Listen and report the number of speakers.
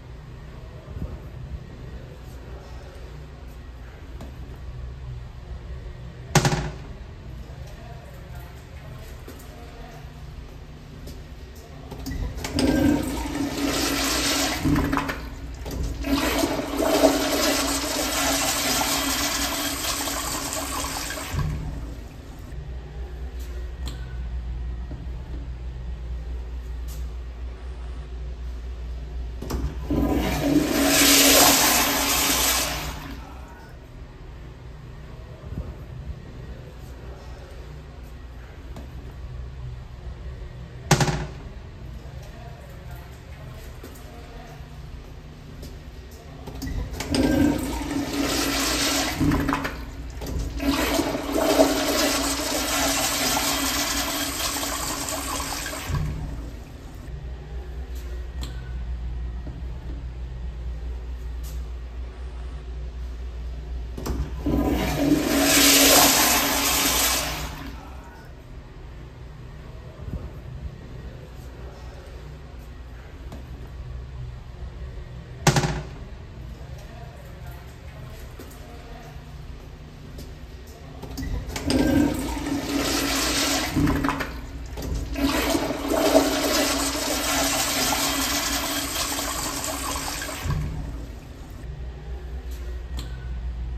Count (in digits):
0